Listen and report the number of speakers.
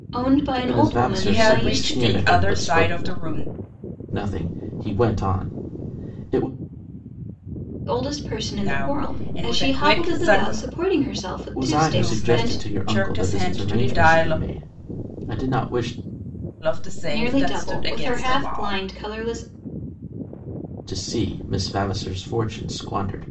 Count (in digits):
3